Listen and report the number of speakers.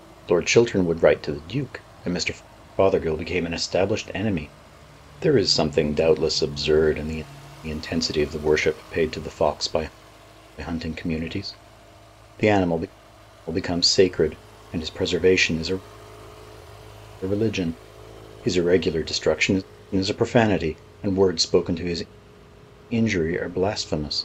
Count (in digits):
1